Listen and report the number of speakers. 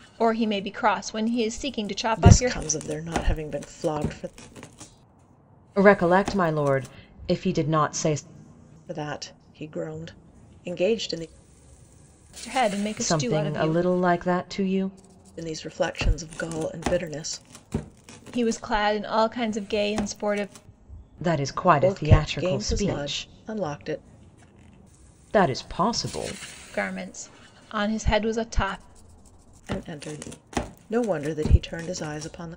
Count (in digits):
3